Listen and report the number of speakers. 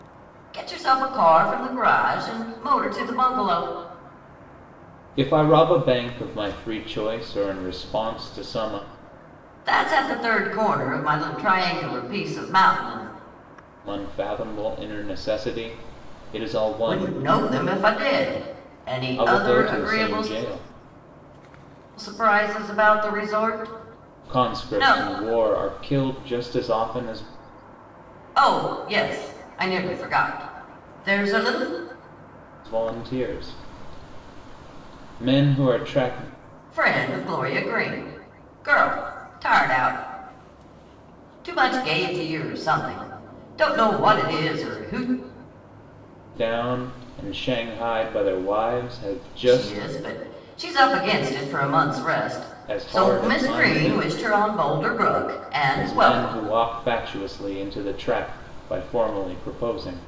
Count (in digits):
2